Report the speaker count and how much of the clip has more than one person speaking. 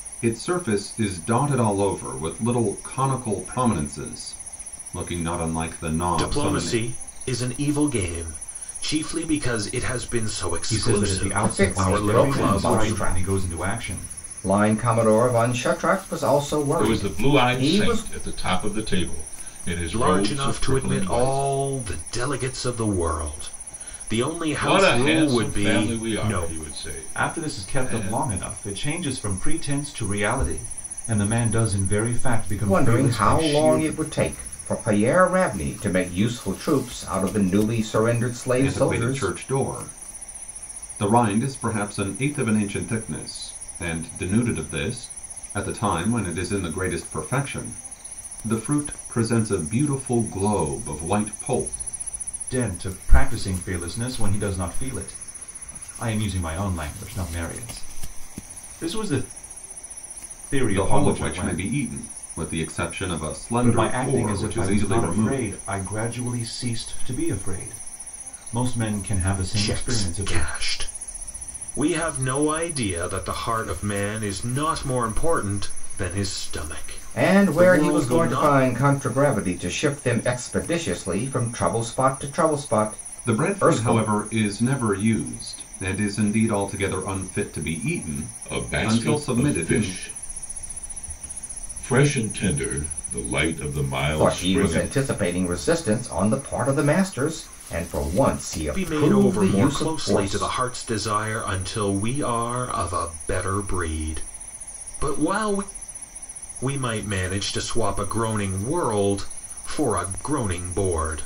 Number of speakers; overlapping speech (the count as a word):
five, about 20%